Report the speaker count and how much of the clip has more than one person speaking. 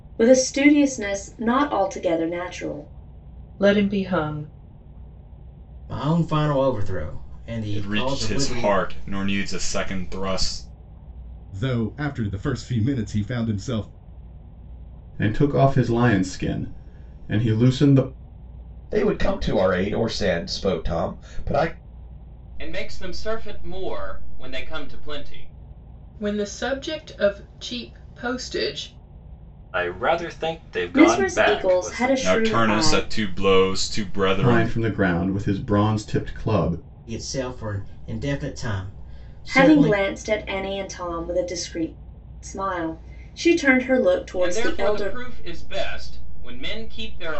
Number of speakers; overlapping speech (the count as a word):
ten, about 11%